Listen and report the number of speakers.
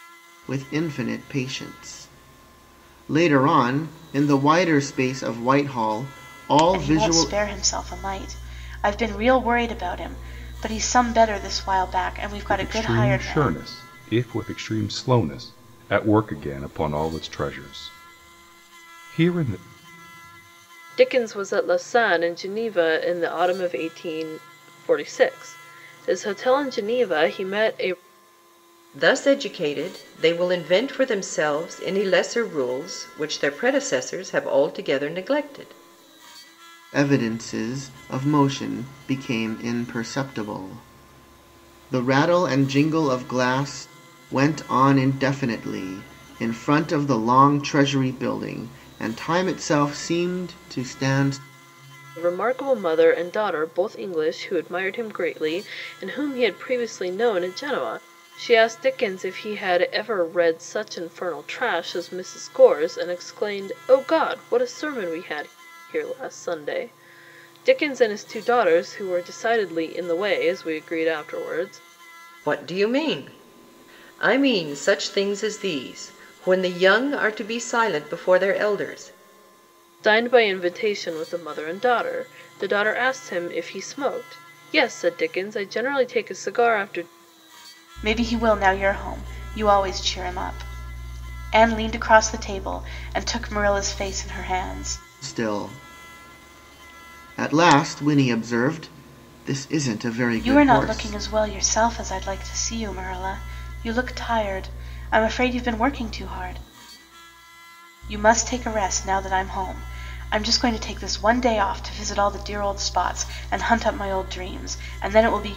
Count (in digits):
5